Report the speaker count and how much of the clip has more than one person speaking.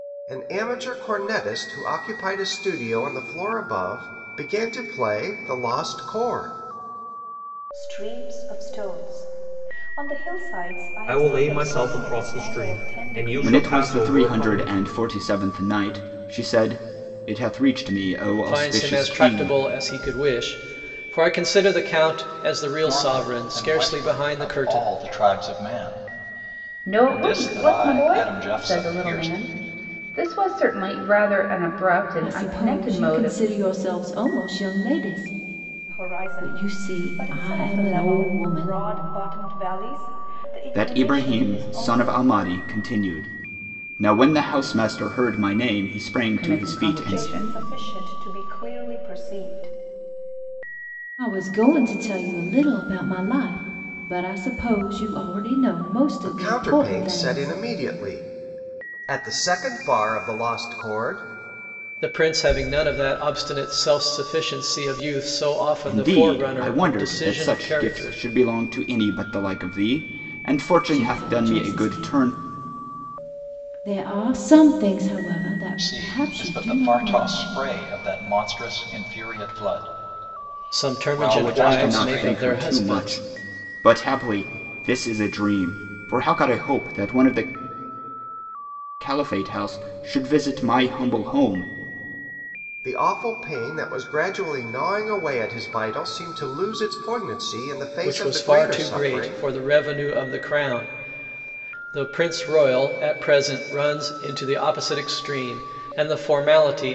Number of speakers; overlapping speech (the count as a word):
eight, about 25%